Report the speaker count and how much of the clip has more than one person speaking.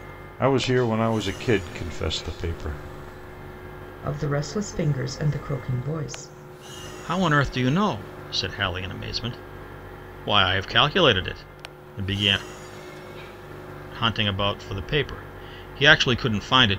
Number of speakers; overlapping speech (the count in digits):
3, no overlap